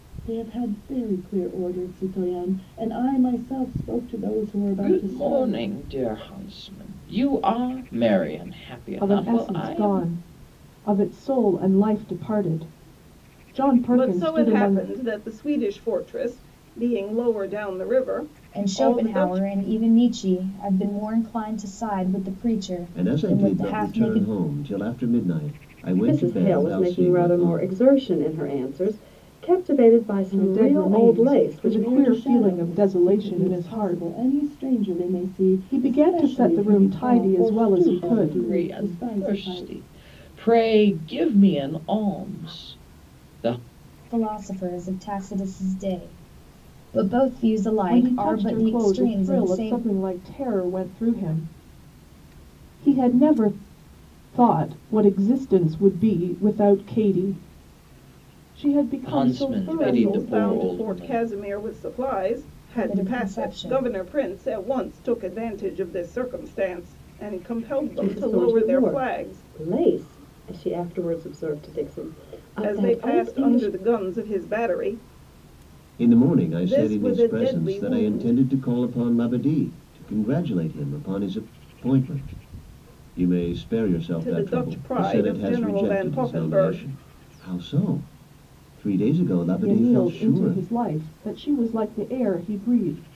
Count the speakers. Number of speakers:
seven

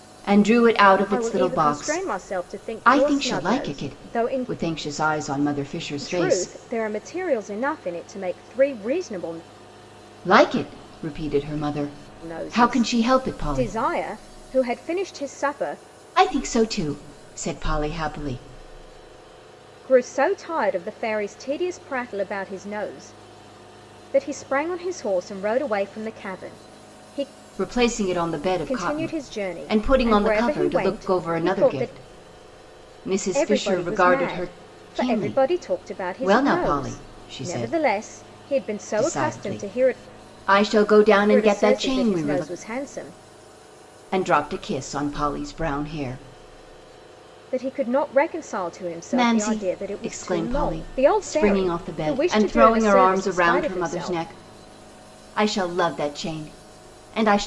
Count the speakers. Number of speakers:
two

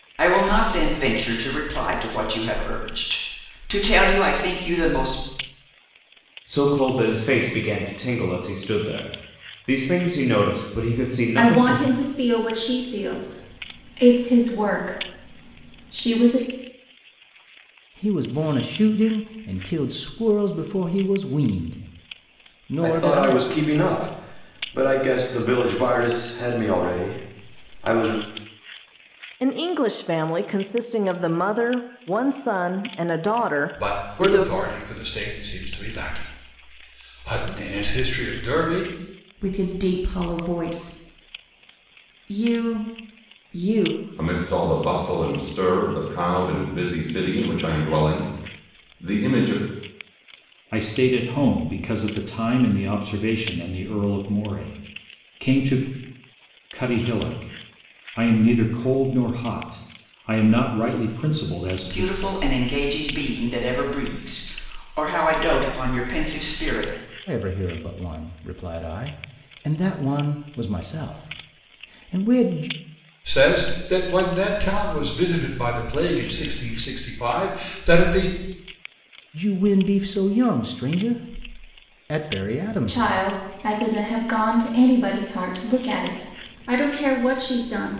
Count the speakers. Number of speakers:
ten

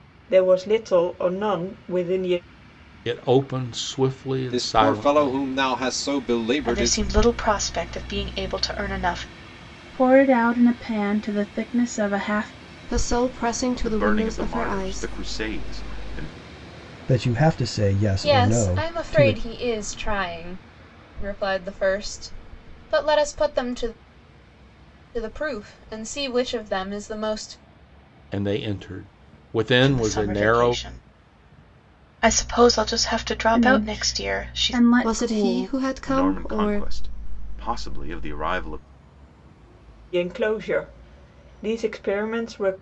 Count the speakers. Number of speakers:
nine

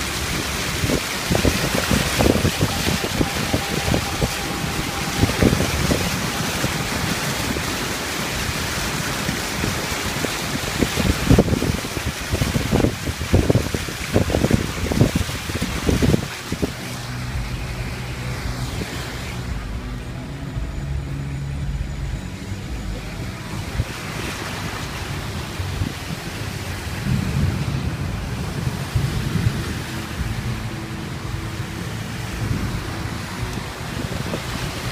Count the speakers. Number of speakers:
zero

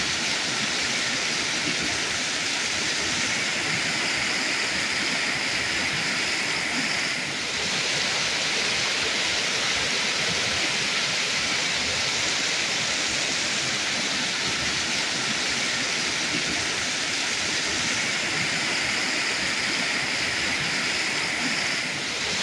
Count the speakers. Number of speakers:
zero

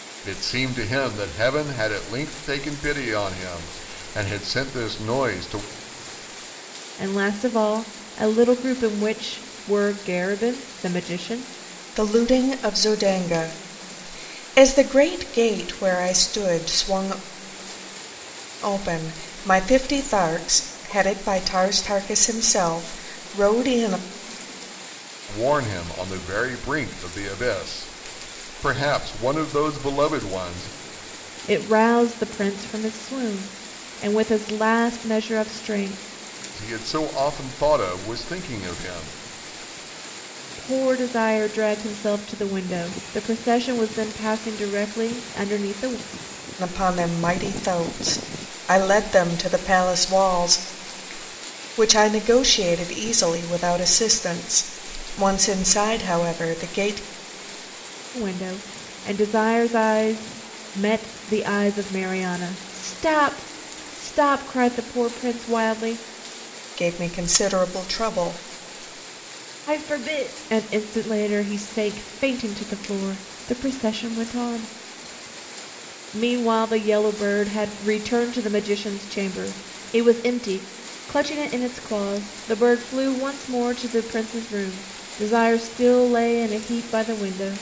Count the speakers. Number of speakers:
three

